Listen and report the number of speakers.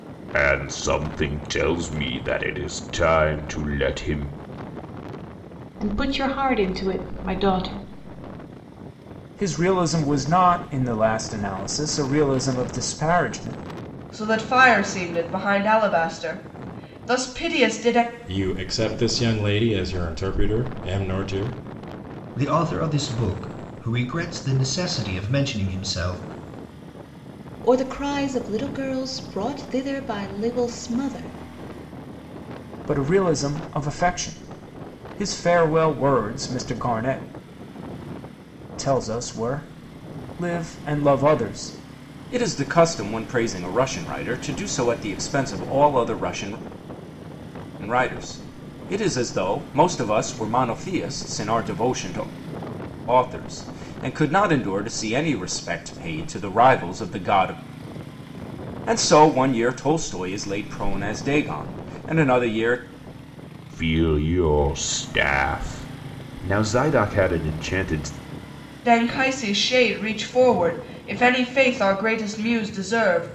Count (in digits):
7